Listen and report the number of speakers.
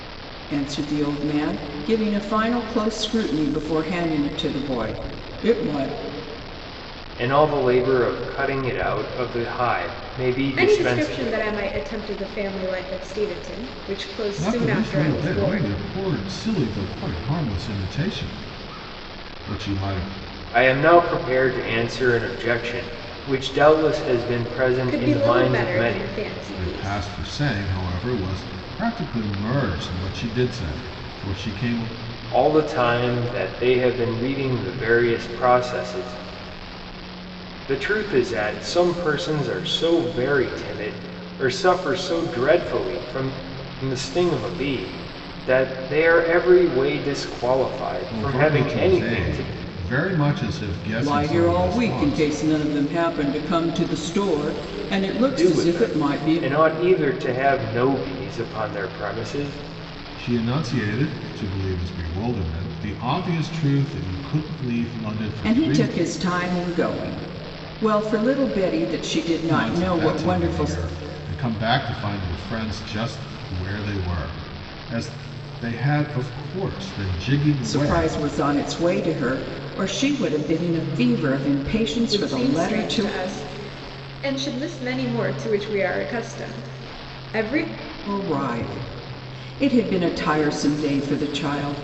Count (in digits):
4